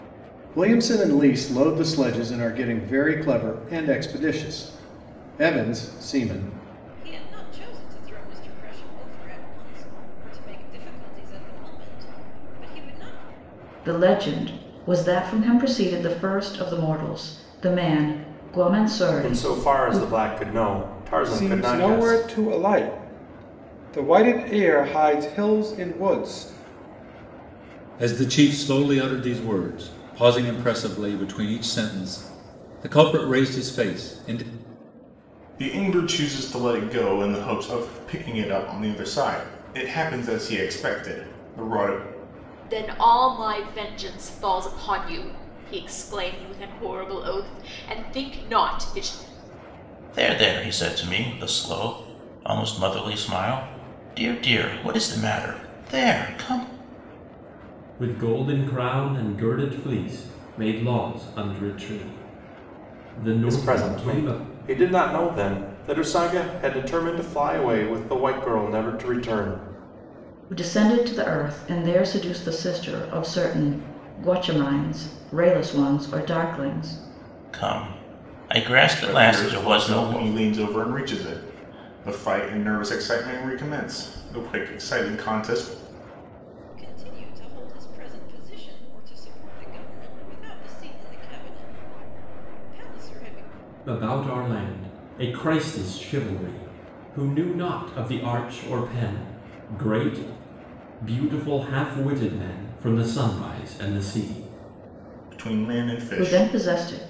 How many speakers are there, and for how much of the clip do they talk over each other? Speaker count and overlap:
ten, about 4%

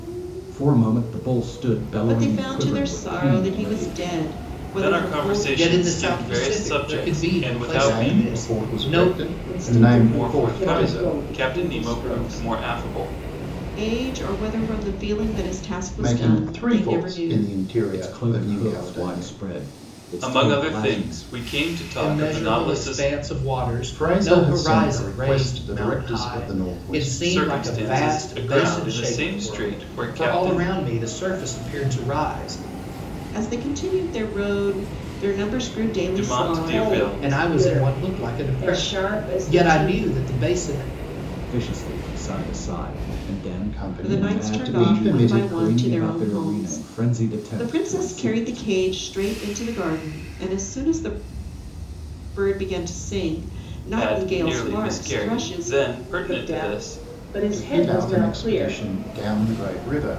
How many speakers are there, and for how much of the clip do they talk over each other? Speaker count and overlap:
six, about 56%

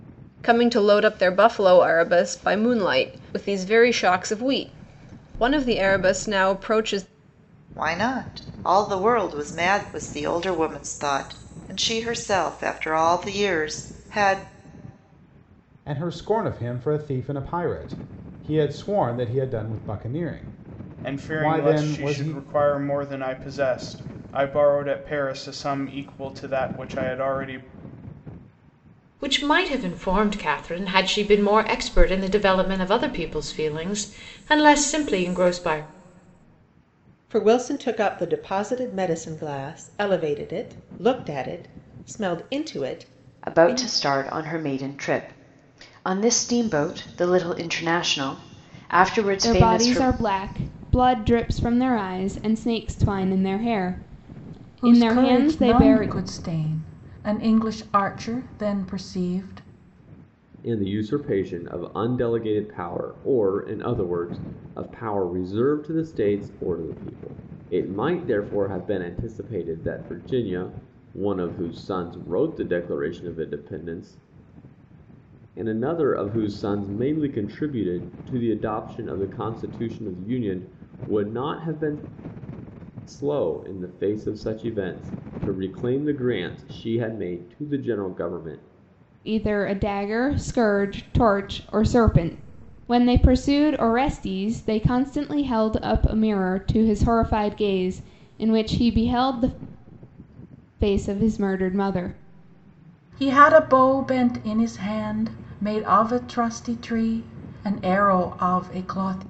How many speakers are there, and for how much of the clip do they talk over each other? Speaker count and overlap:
ten, about 4%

